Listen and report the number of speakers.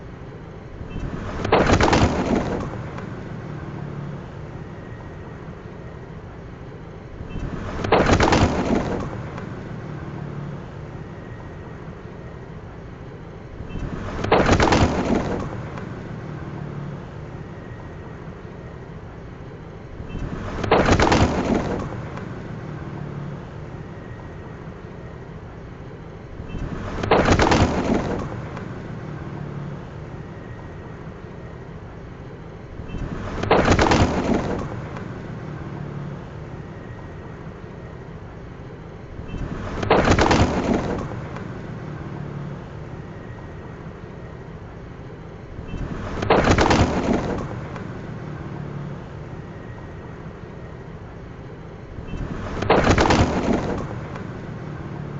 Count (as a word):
zero